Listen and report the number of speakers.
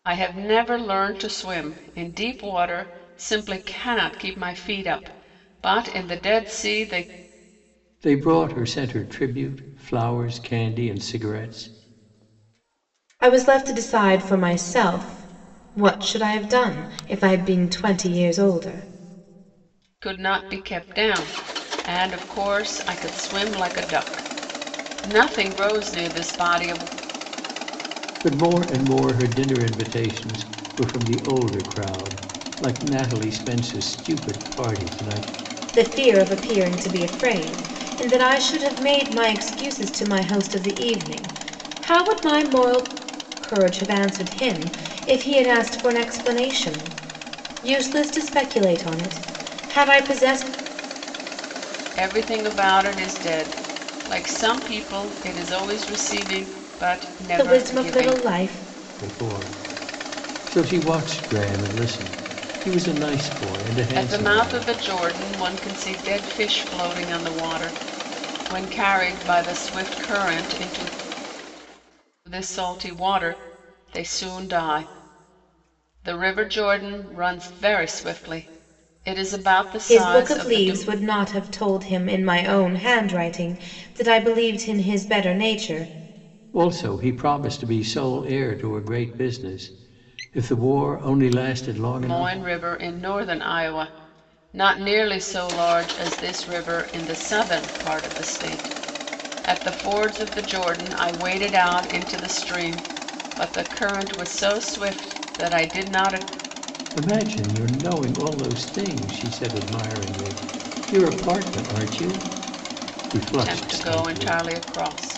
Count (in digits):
3